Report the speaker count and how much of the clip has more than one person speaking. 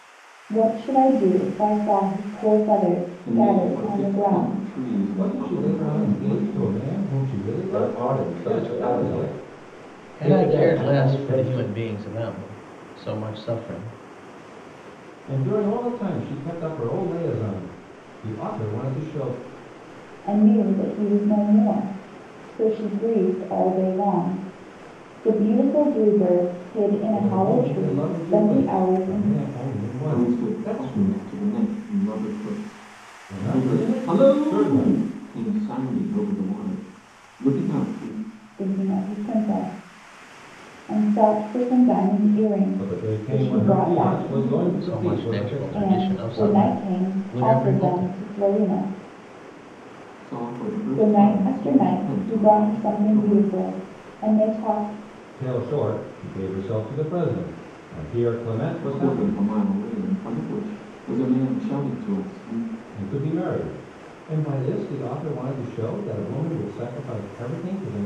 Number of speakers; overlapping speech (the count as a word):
five, about 30%